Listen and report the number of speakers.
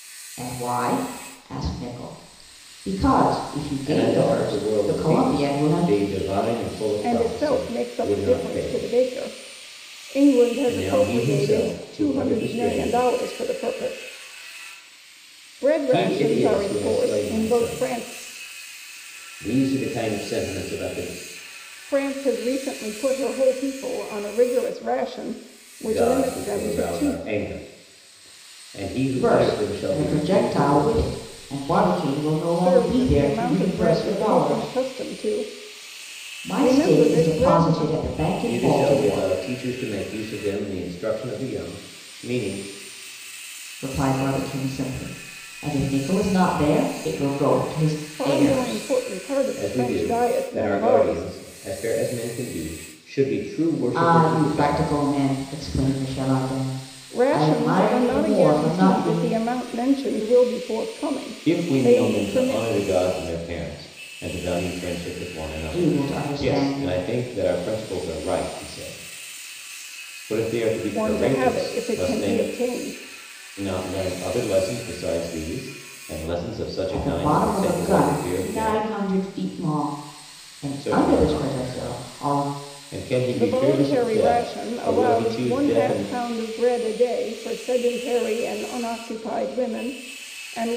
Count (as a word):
three